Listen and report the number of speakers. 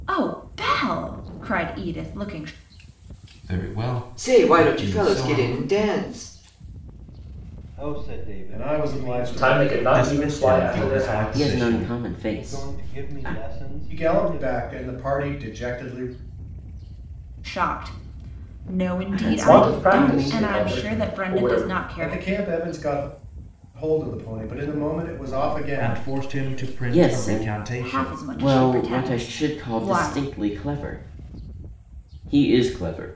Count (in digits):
8